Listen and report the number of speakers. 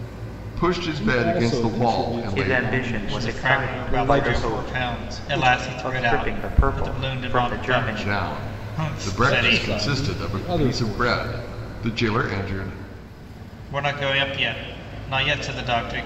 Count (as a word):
four